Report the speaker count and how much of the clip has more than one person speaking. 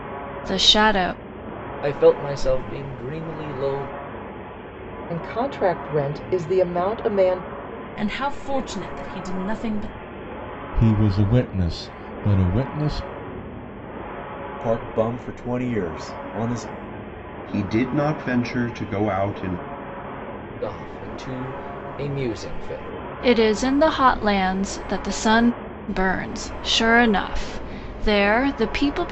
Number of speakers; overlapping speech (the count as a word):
seven, no overlap